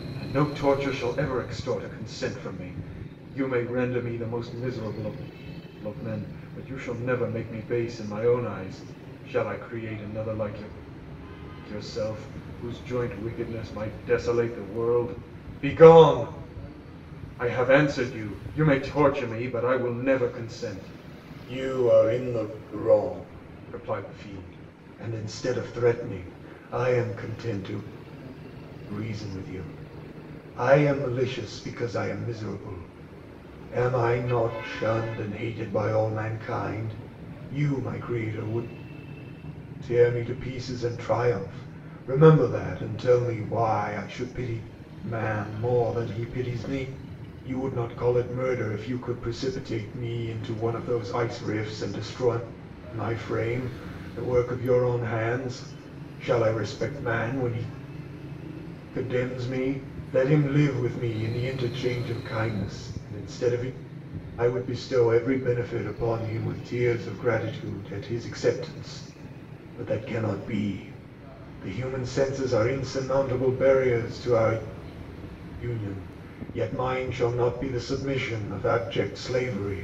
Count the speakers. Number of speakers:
one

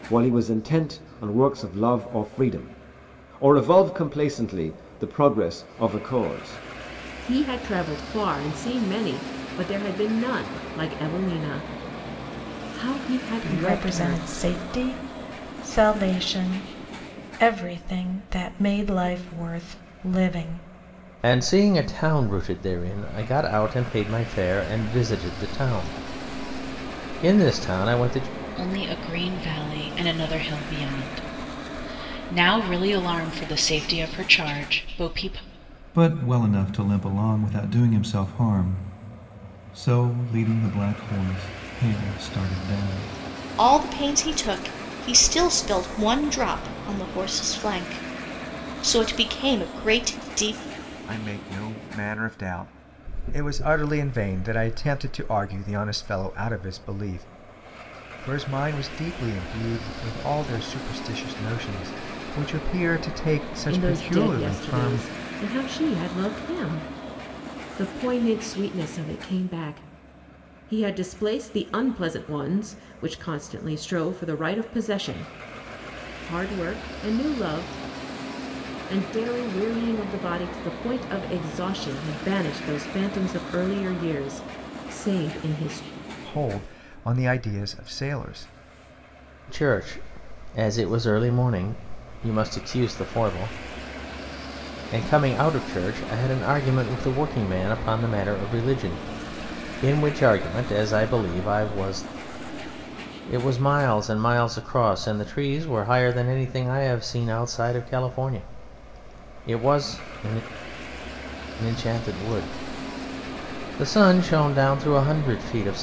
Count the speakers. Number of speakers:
eight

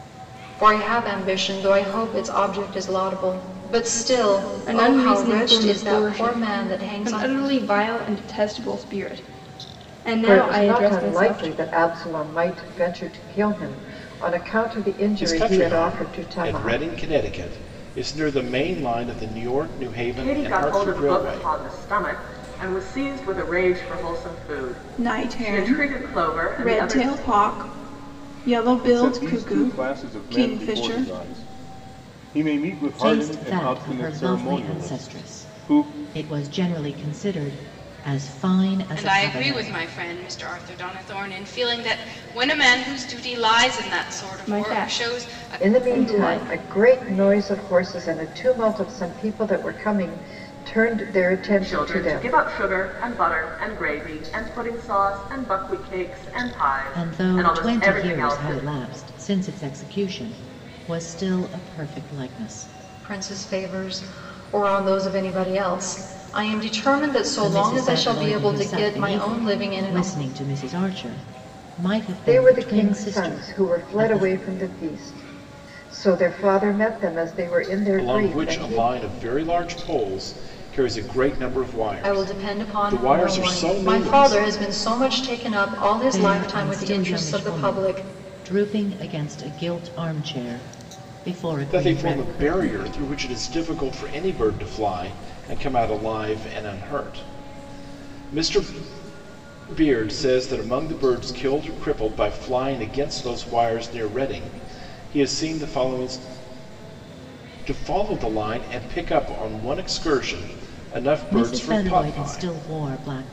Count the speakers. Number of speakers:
nine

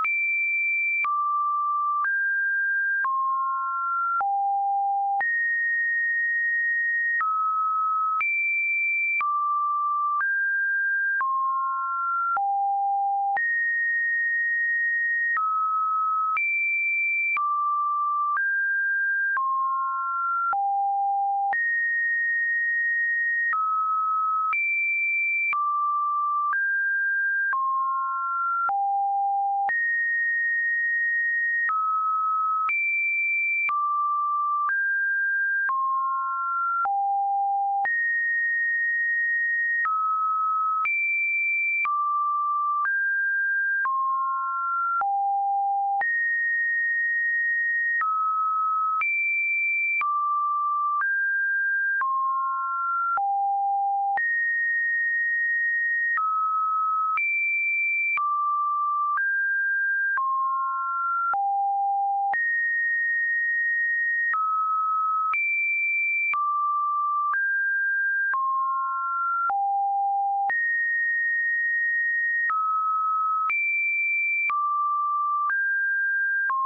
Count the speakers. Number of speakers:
zero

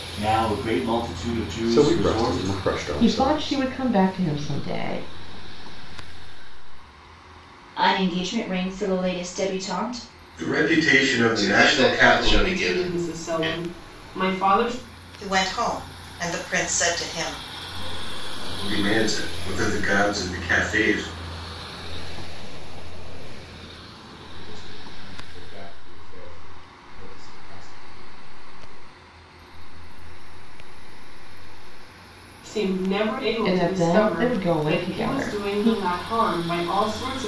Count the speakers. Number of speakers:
ten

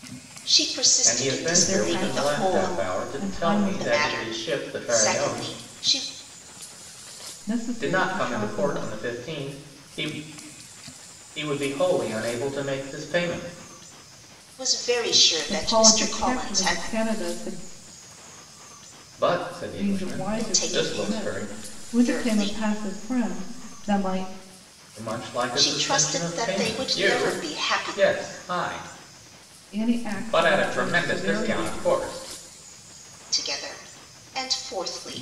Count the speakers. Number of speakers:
three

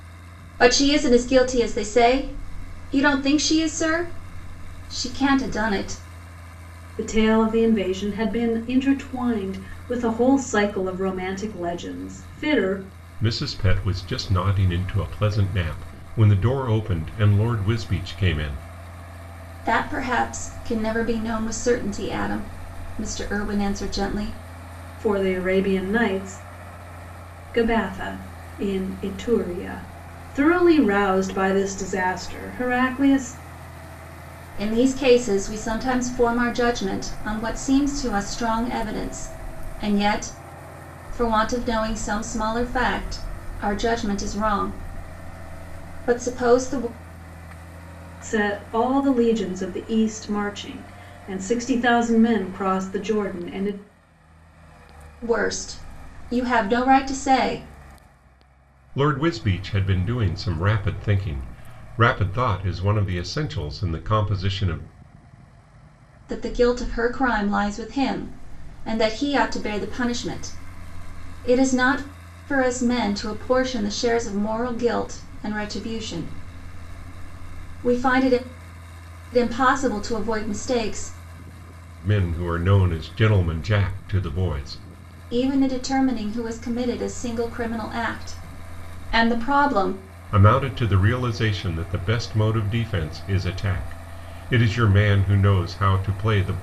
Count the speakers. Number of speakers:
three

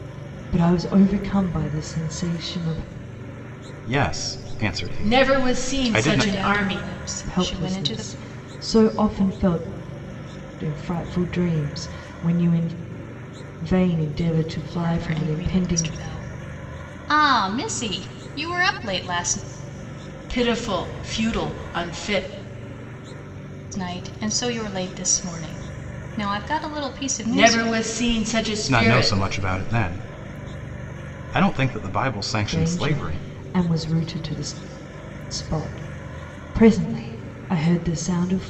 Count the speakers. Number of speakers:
four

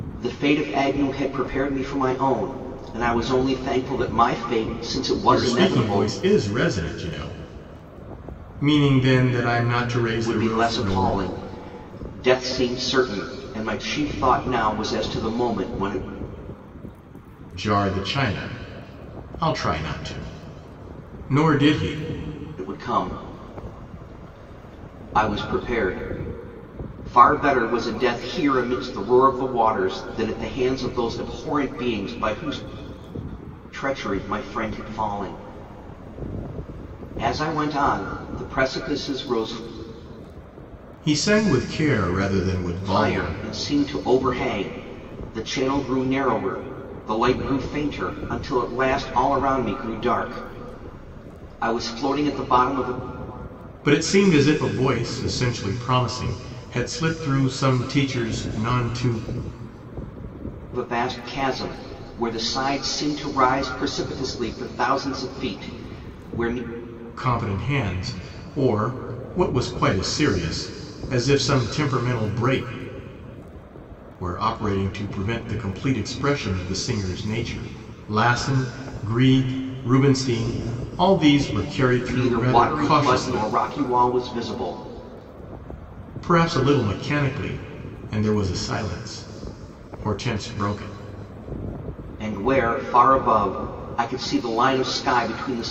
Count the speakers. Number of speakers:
two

